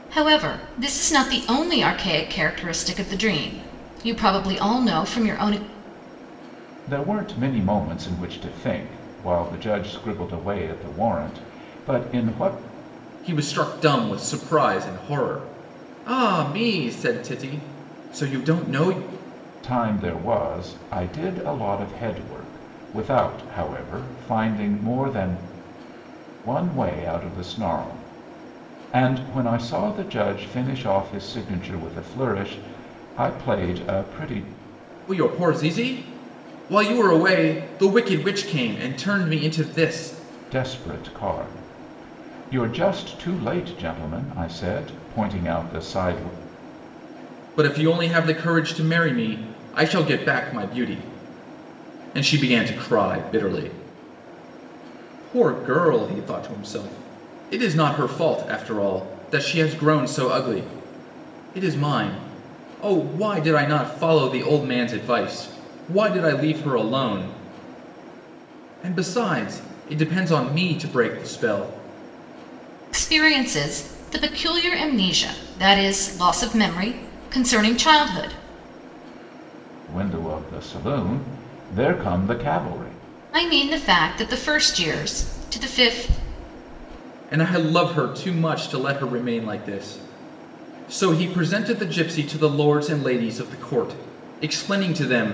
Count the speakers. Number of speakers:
3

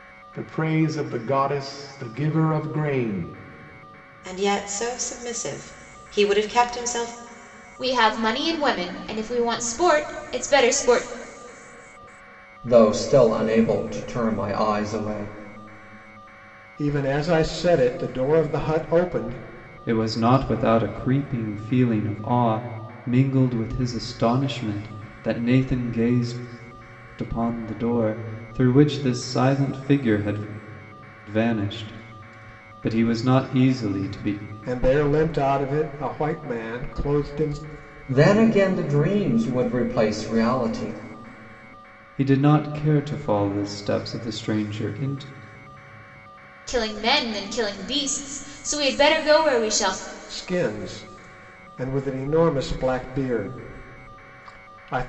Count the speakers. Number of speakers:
6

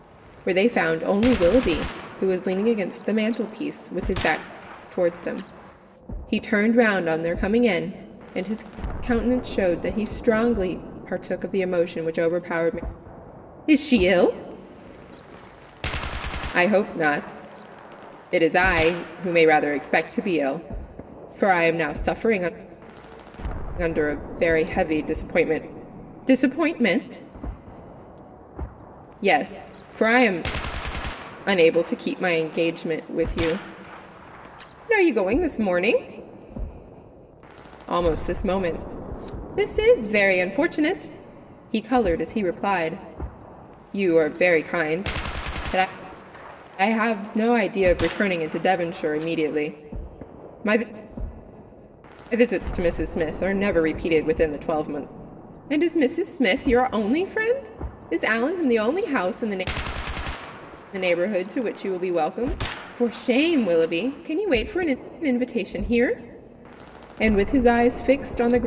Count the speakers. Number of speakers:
1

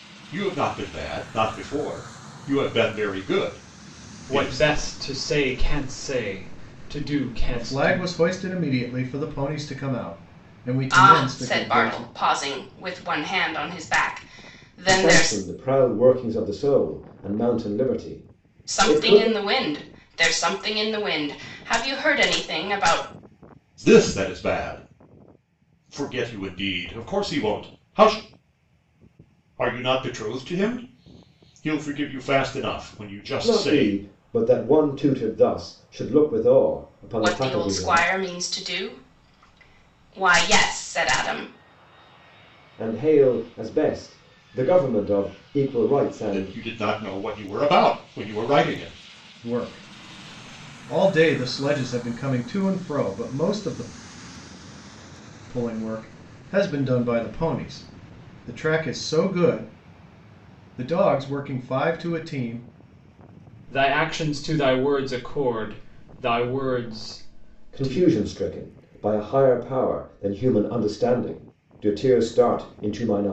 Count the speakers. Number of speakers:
5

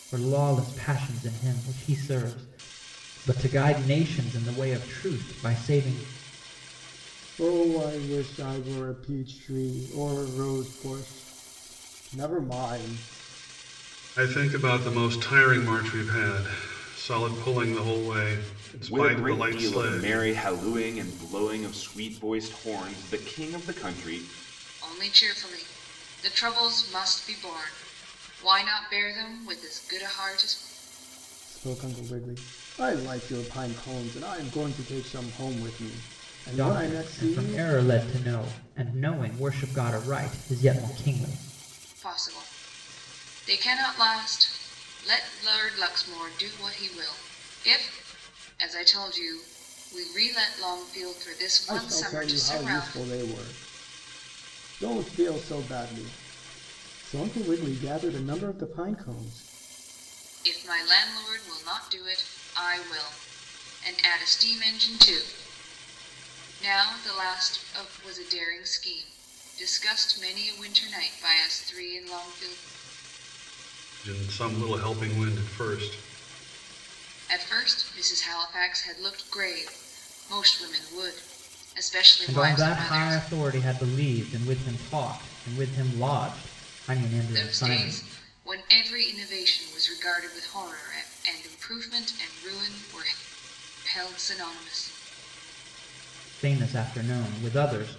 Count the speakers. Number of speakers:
5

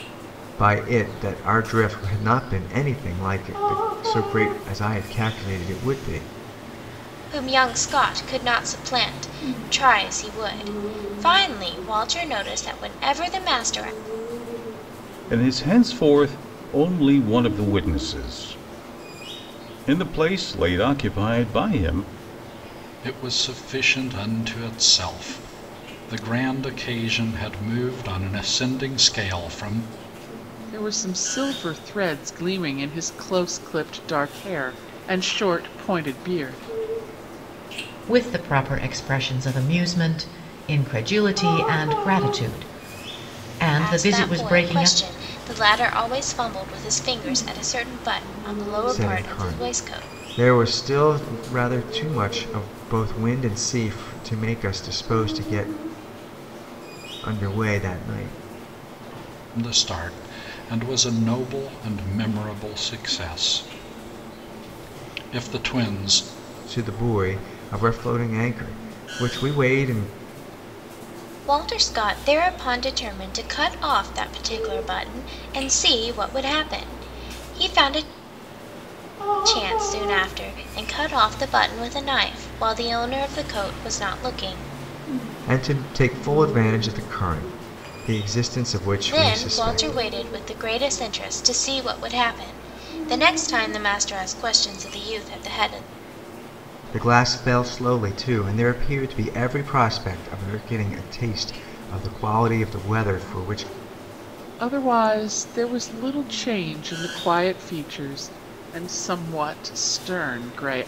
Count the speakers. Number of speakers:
6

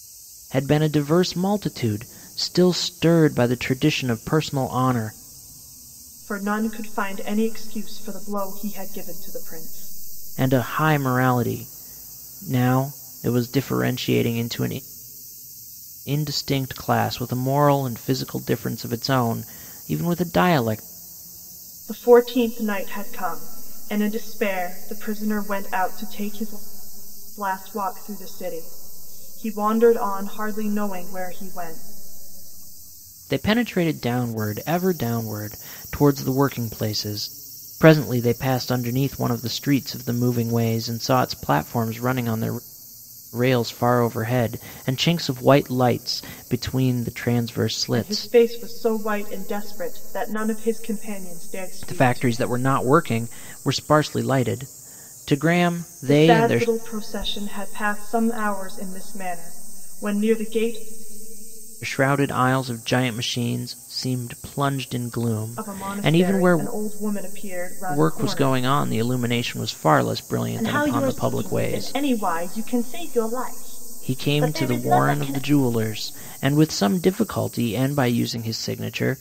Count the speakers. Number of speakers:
2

